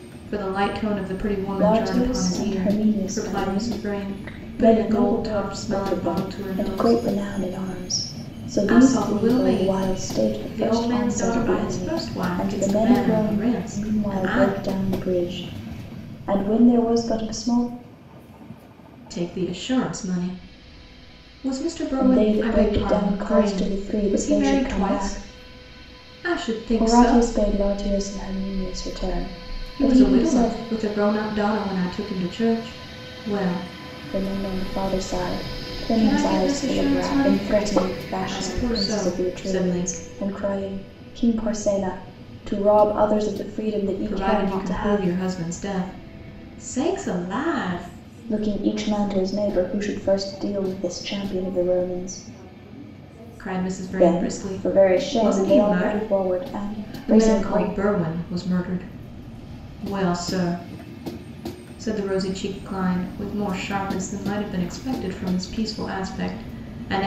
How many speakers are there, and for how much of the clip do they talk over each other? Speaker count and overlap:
2, about 34%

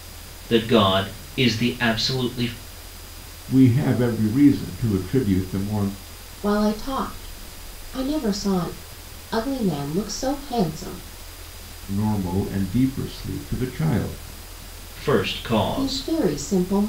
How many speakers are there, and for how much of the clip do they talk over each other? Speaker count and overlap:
3, about 3%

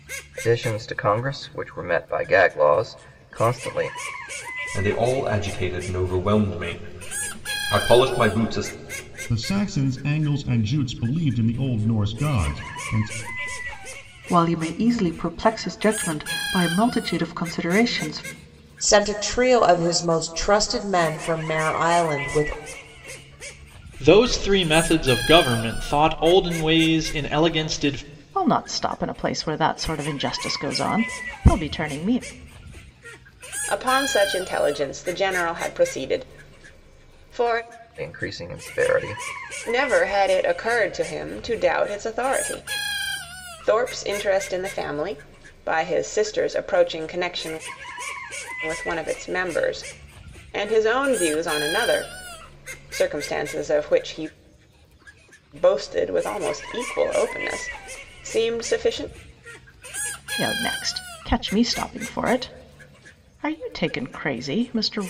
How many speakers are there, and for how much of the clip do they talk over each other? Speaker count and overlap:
8, no overlap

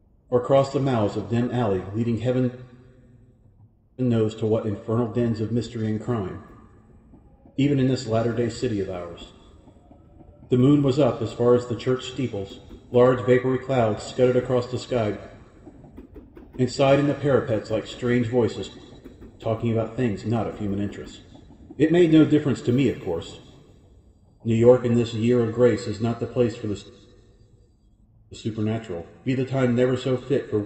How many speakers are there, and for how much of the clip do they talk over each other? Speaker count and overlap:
1, no overlap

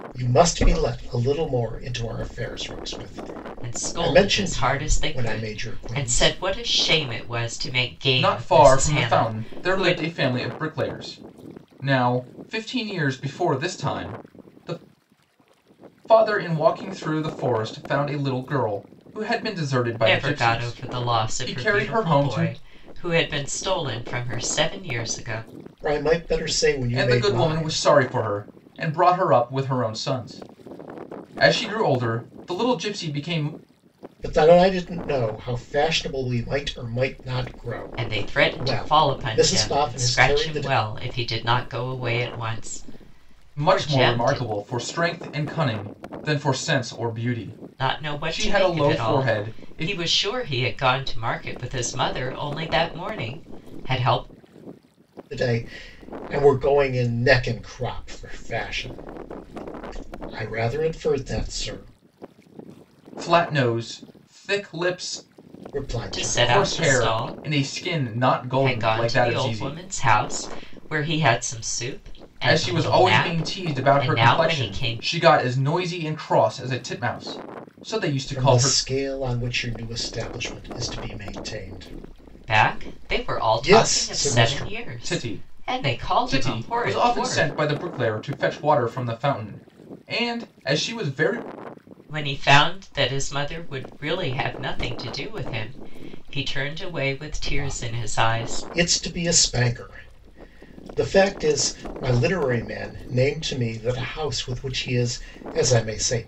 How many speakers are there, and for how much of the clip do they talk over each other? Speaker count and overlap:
3, about 24%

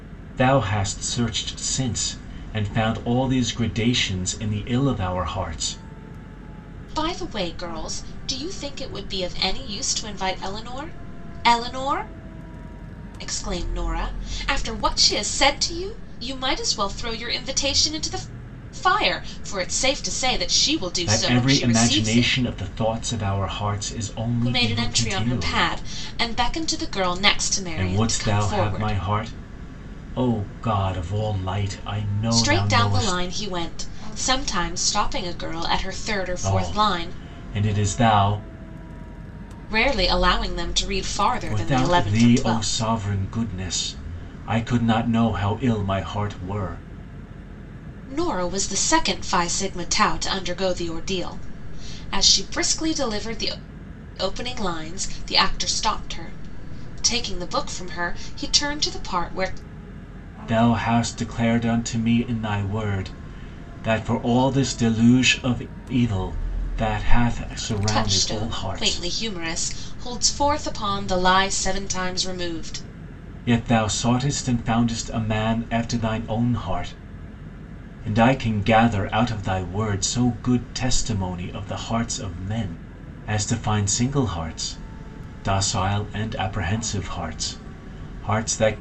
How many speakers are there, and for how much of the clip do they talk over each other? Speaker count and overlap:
2, about 9%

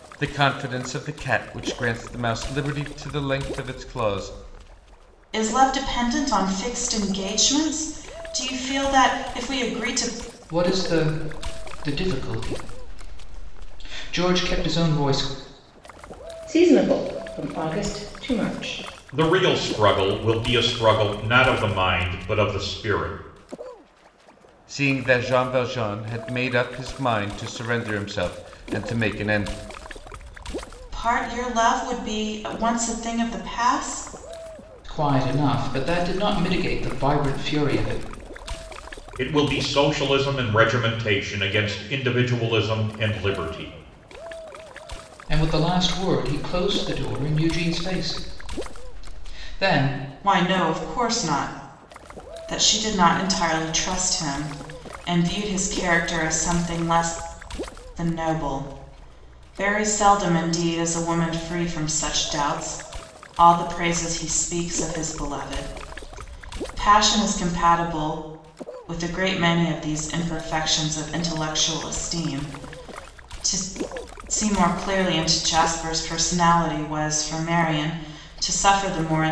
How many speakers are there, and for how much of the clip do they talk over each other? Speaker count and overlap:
5, no overlap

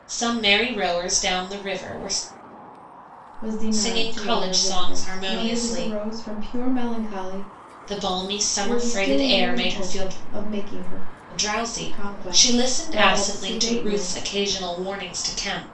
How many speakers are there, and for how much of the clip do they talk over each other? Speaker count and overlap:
2, about 39%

